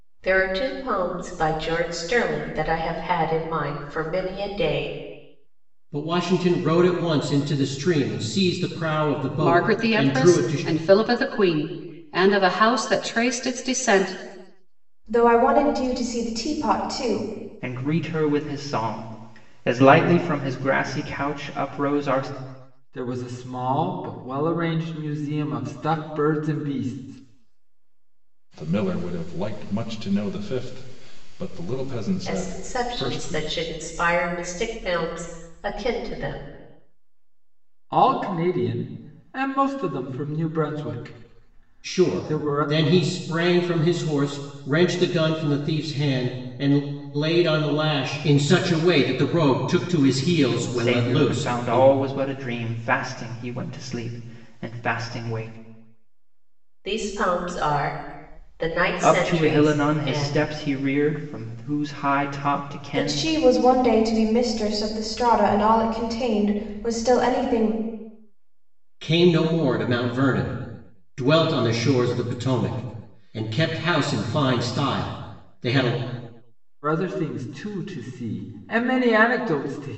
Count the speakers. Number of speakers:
7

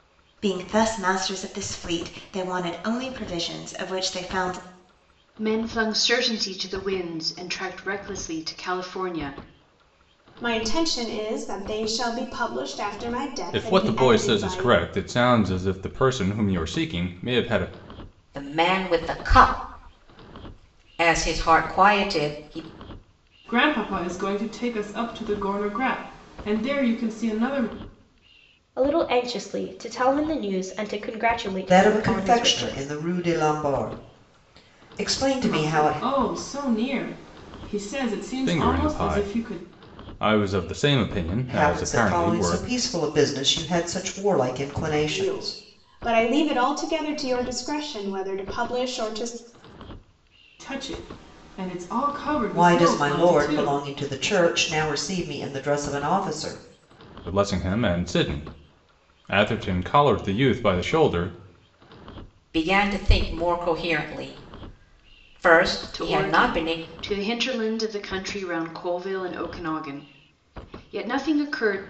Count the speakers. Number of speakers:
8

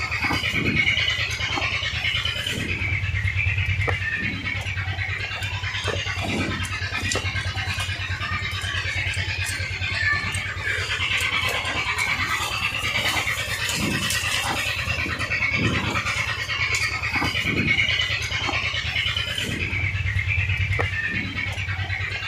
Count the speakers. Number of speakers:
0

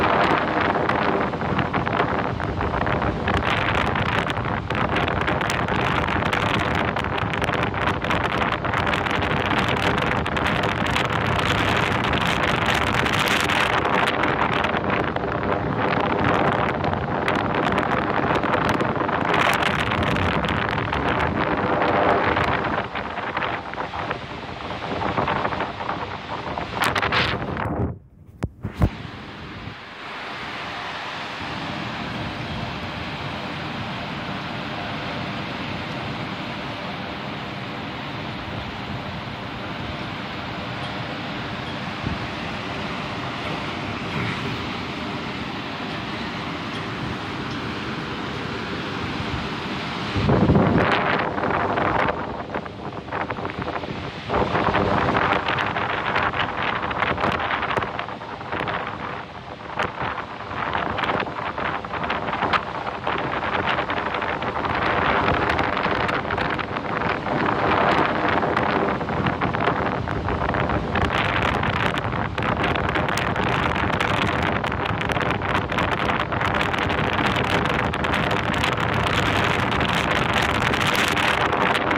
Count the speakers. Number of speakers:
0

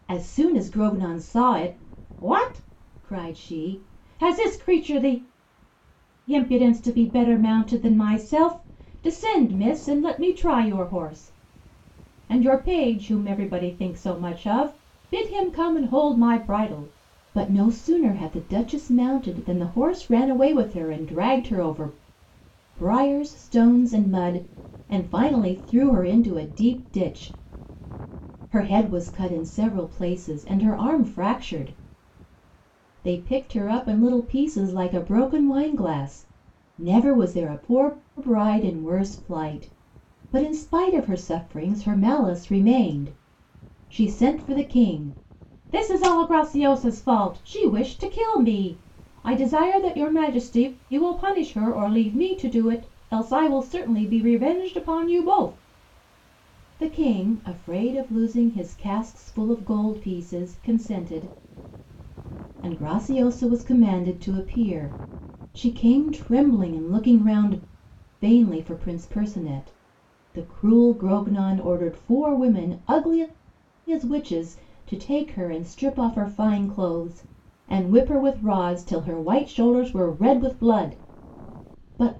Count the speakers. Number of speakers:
1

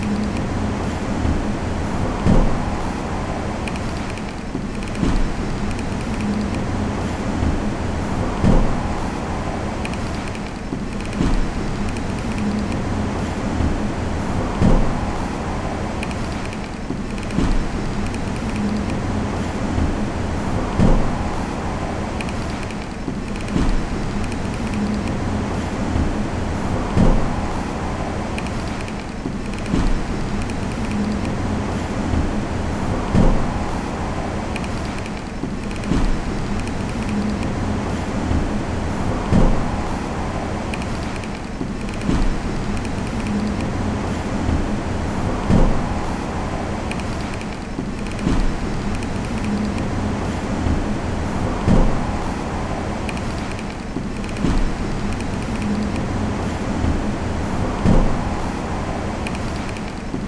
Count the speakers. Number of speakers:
0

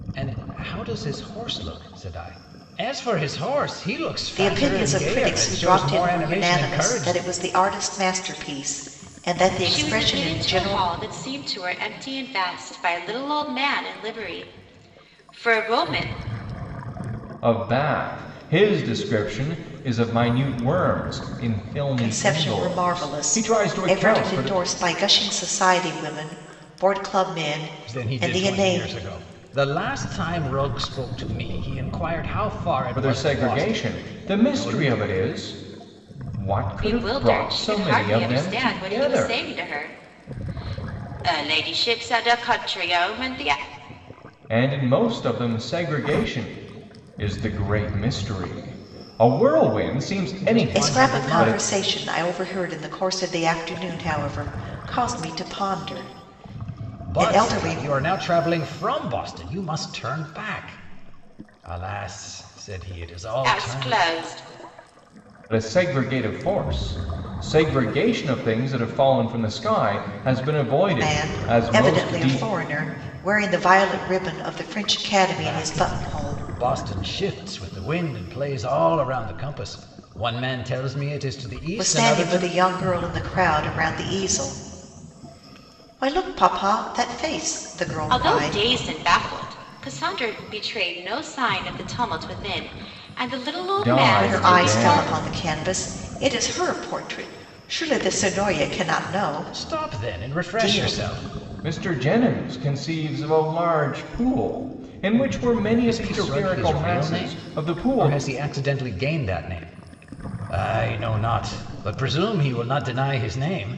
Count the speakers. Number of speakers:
4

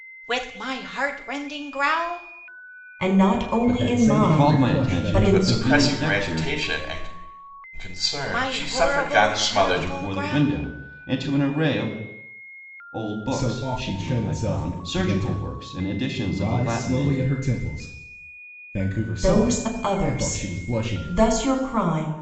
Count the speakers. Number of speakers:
5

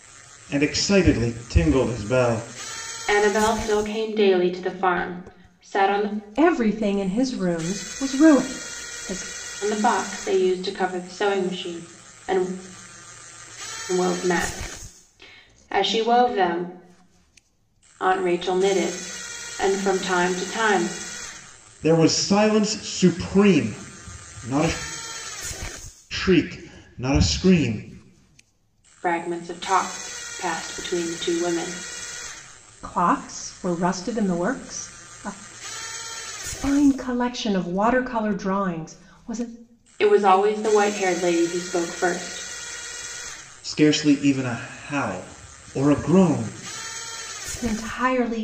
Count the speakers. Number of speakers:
3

